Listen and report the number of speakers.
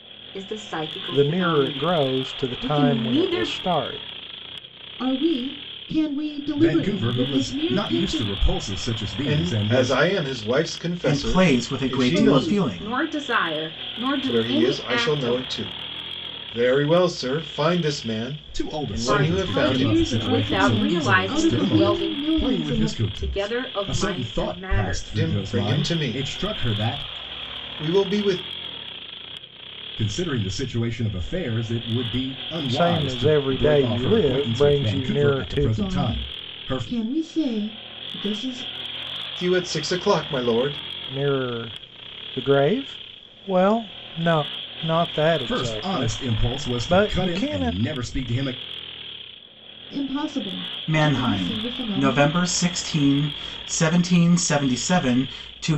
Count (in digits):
6